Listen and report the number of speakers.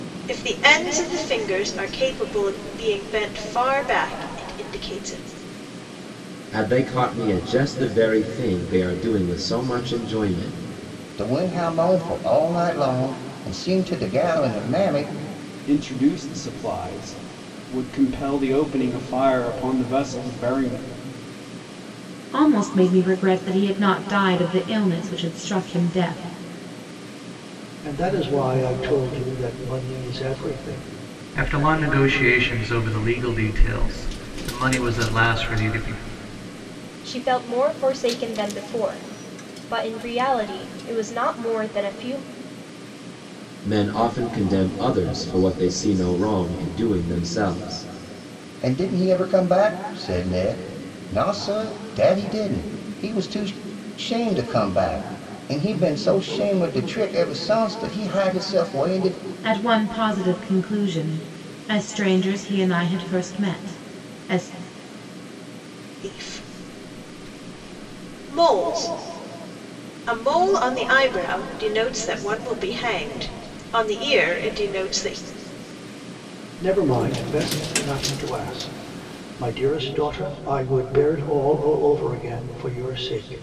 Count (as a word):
eight